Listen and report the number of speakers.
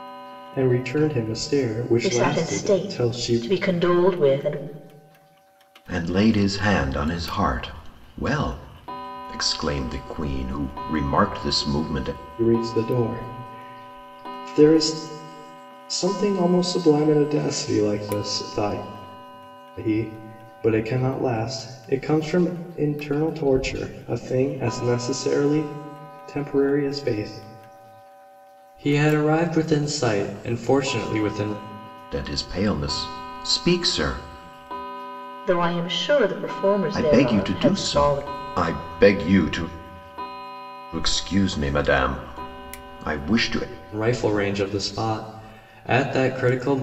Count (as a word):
three